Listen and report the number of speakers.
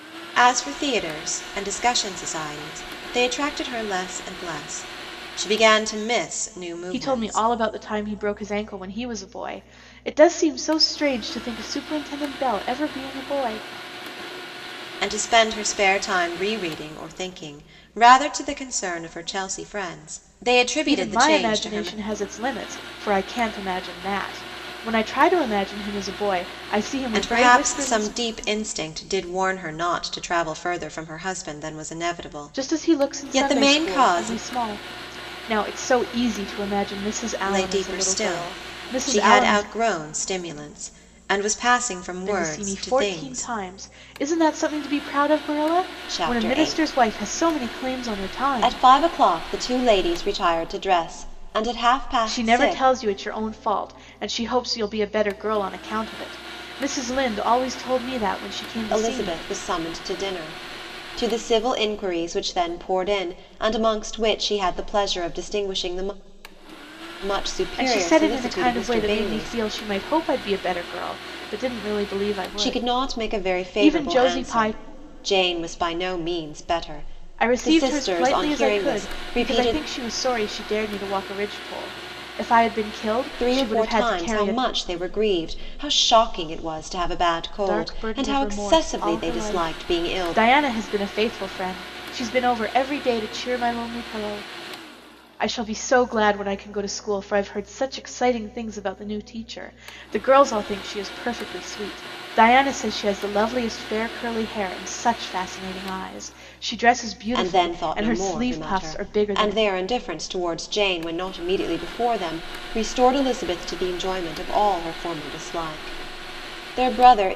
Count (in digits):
2